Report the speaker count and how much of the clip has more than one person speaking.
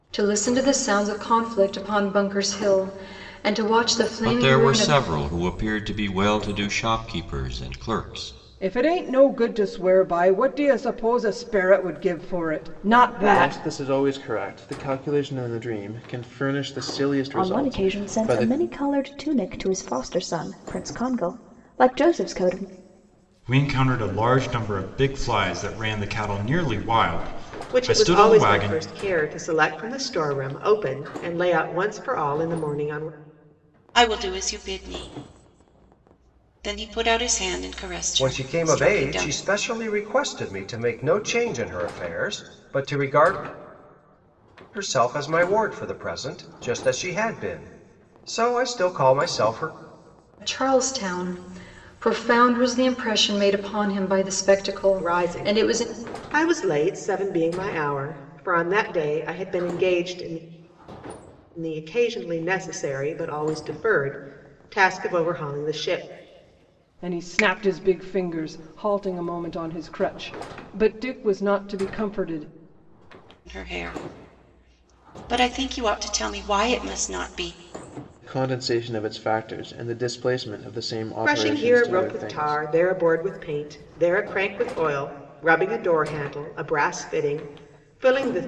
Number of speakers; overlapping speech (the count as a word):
nine, about 8%